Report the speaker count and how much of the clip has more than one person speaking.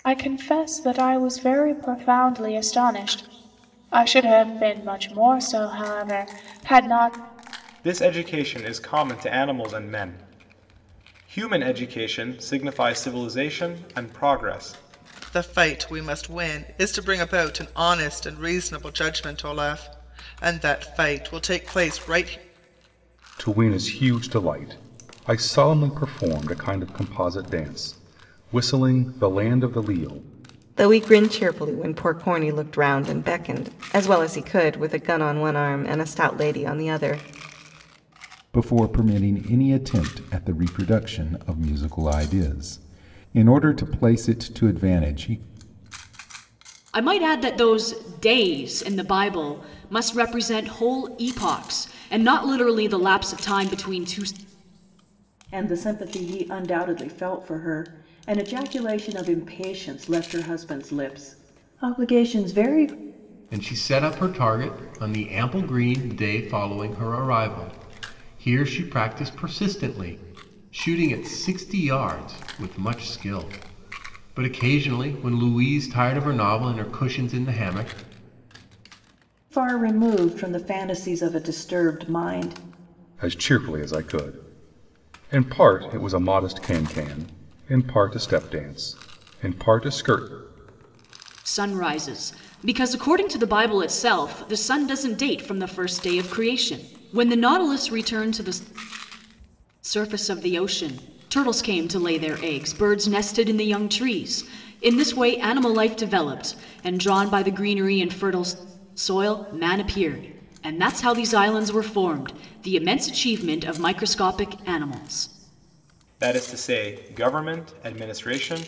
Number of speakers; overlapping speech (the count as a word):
nine, no overlap